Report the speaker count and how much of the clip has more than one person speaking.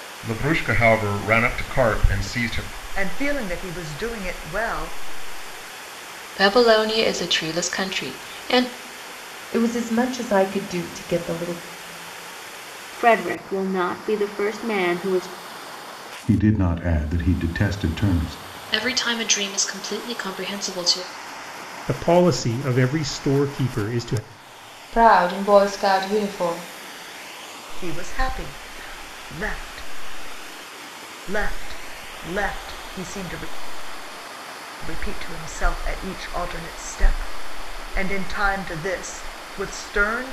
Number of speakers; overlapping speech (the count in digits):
9, no overlap